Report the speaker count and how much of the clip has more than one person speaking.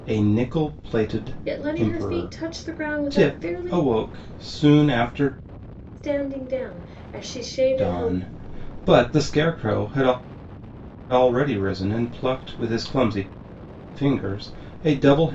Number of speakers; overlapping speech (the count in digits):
2, about 14%